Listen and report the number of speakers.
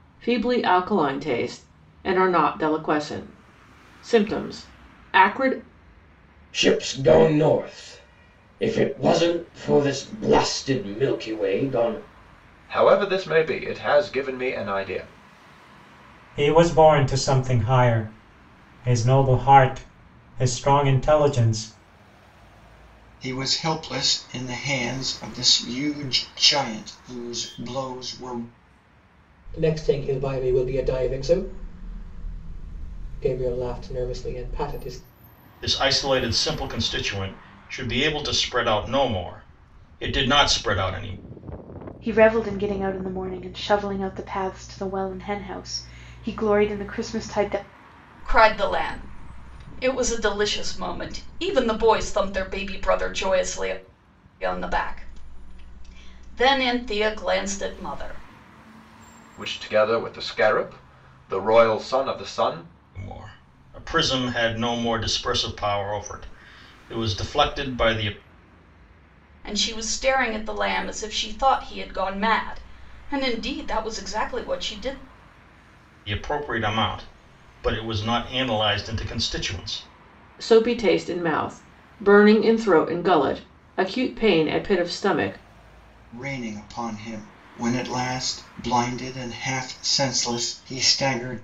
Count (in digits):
9